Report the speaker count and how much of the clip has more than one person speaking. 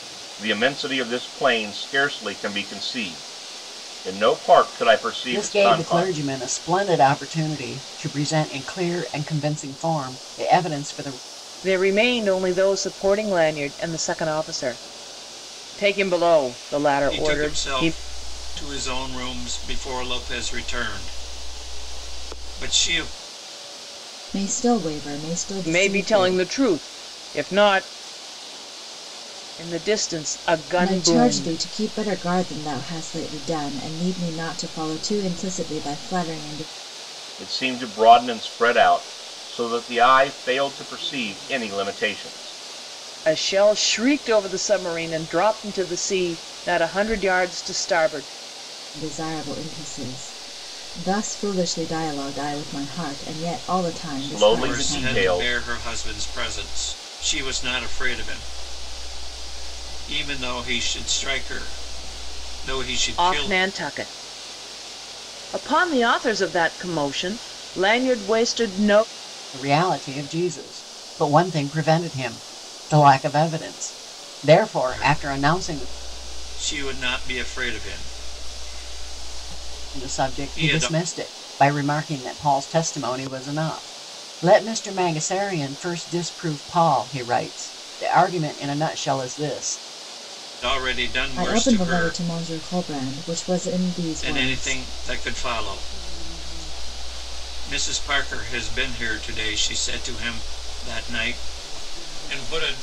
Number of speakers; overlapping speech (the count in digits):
5, about 9%